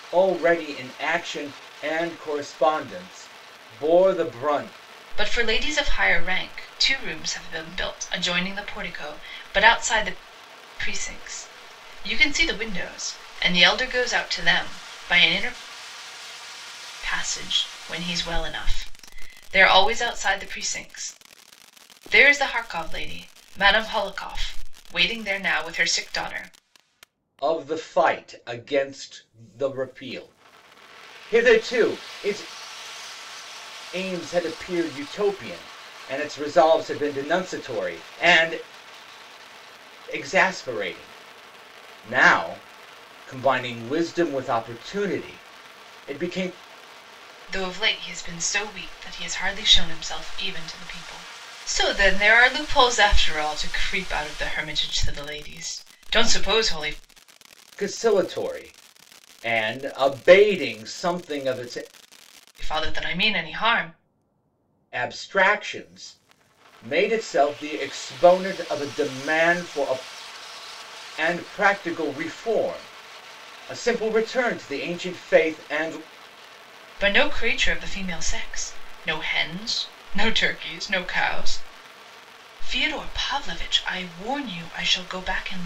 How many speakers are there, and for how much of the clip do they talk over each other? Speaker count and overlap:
2, no overlap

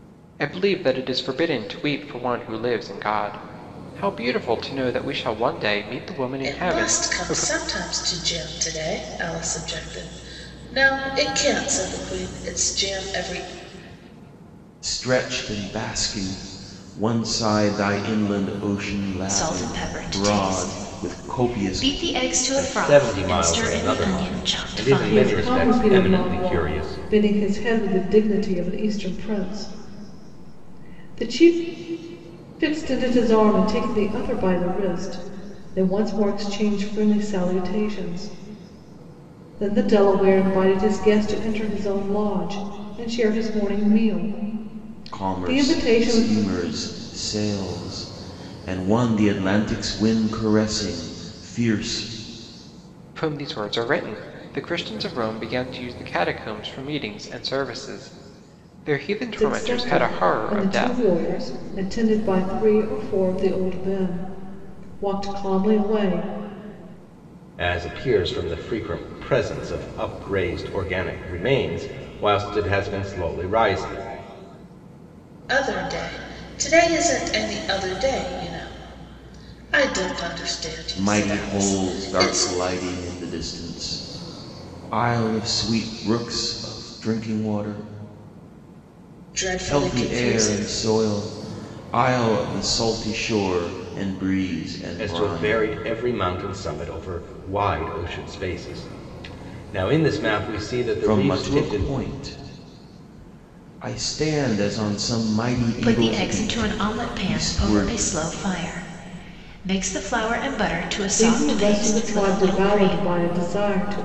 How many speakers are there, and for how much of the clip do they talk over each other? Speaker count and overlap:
6, about 17%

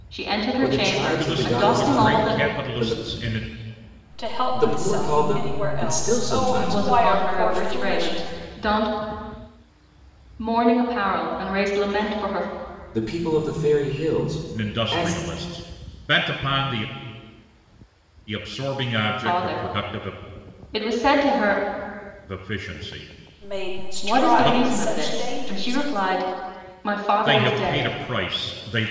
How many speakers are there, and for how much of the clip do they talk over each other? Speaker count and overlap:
4, about 38%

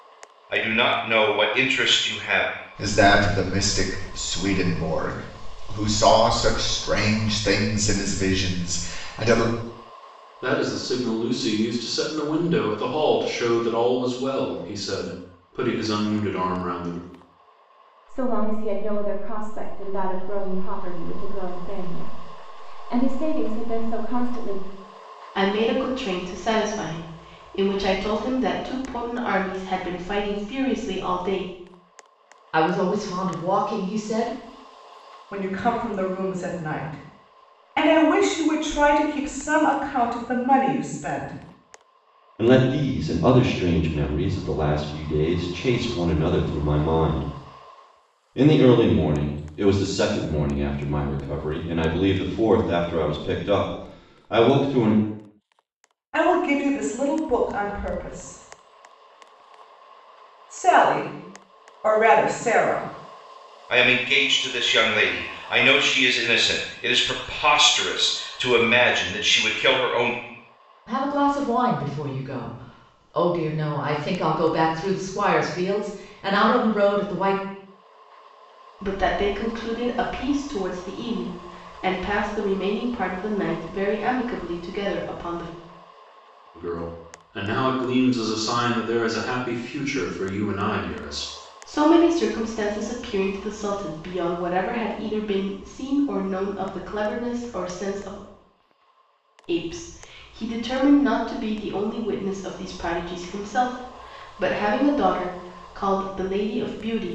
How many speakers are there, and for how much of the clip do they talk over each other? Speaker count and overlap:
8, no overlap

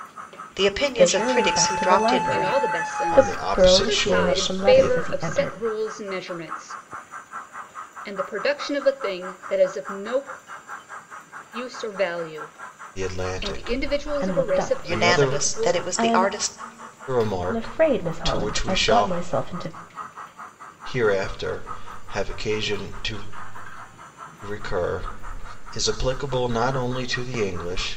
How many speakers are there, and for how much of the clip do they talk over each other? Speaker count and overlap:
4, about 35%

